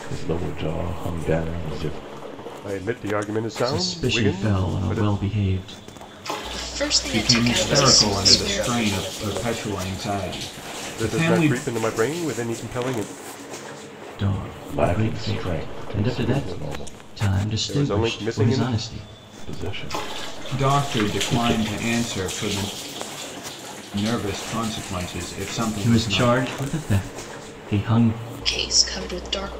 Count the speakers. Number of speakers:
6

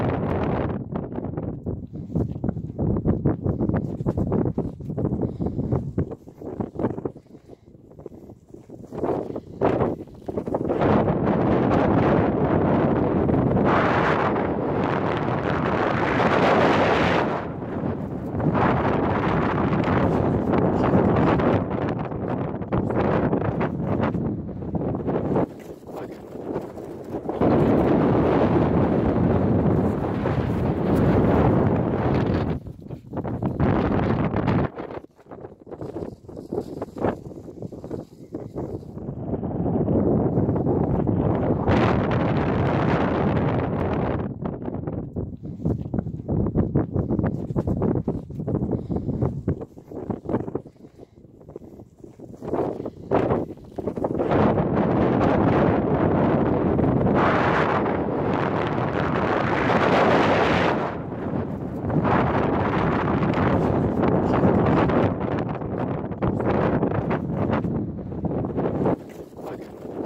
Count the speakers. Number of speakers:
0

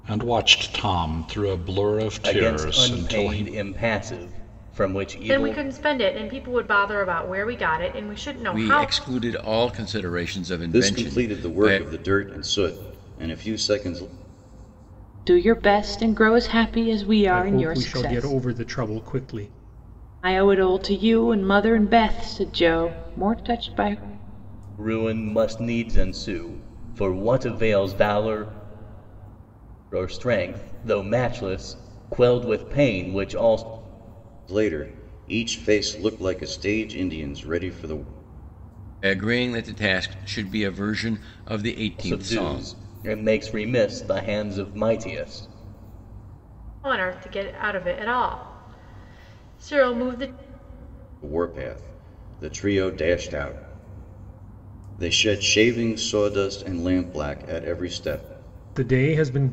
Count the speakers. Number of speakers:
7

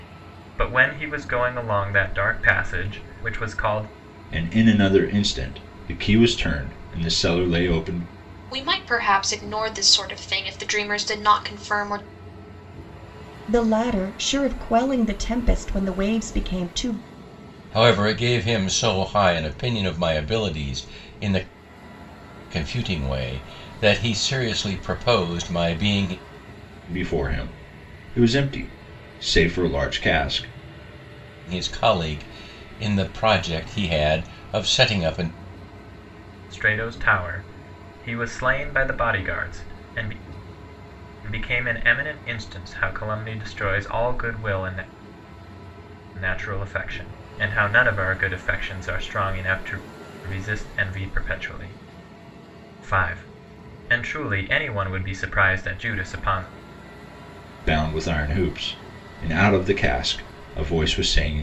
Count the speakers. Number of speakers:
5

